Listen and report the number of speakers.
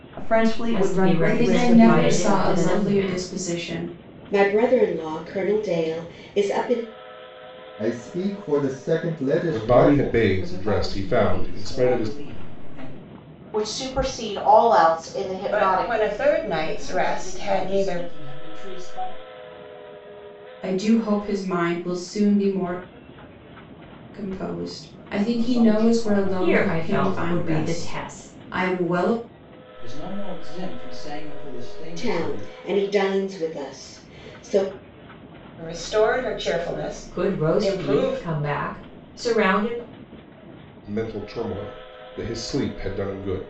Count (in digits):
10